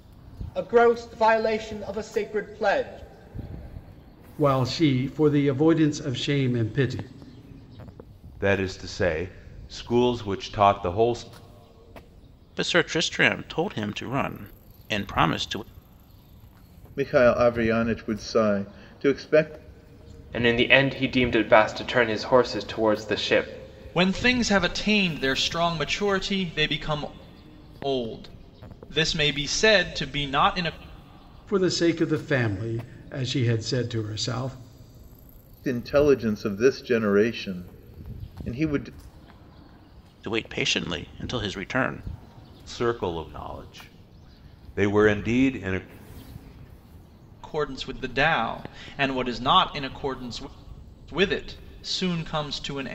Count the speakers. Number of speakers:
7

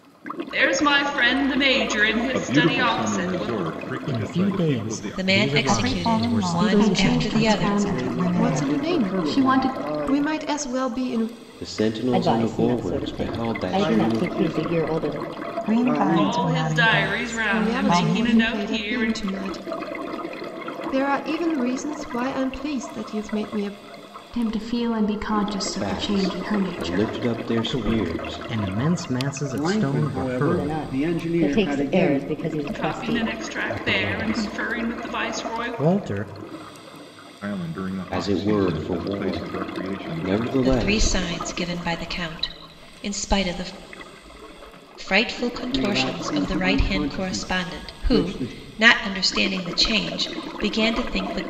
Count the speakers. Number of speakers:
10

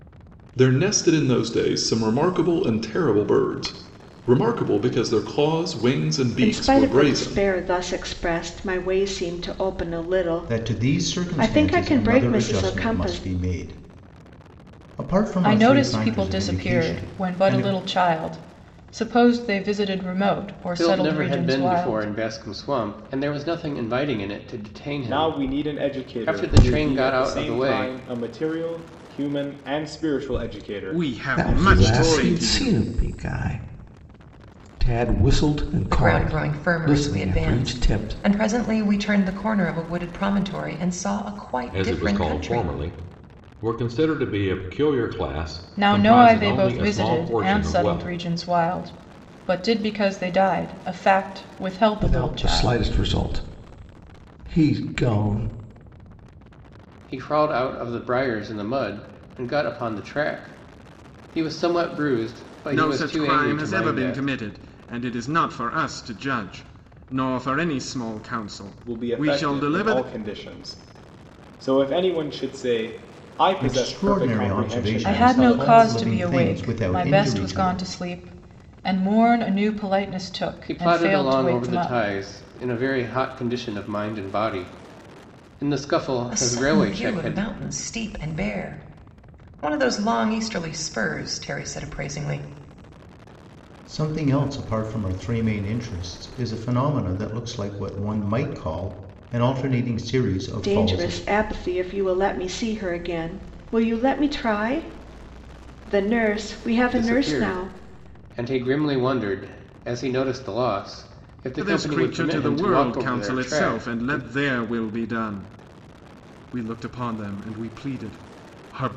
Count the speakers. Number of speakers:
10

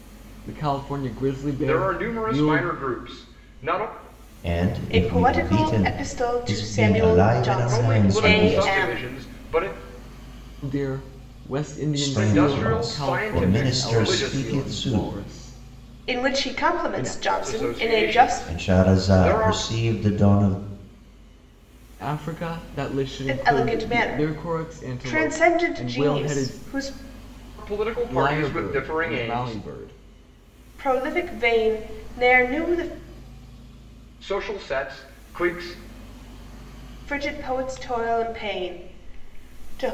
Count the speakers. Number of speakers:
4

